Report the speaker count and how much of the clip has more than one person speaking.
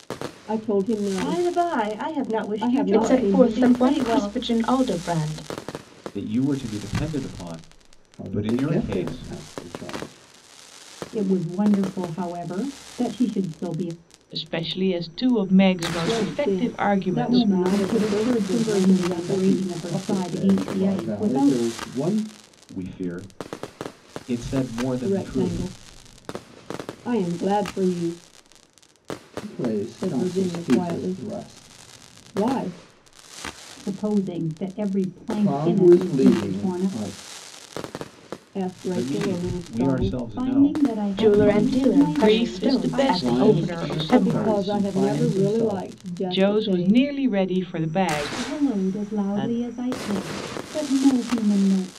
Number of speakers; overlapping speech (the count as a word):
seven, about 45%